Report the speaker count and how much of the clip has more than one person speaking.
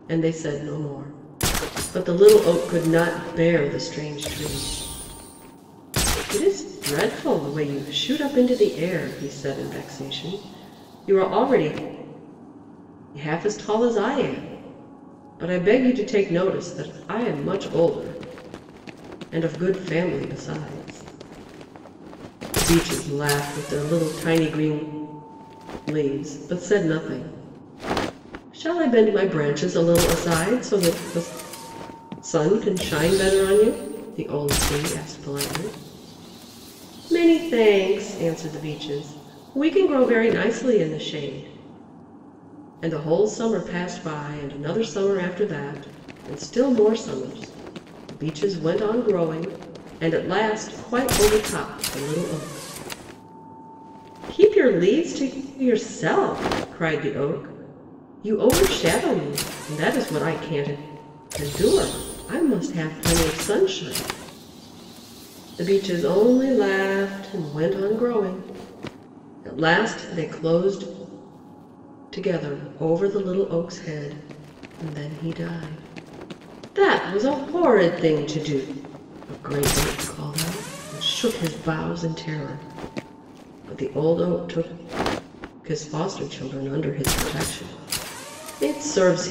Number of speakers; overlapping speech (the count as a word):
one, no overlap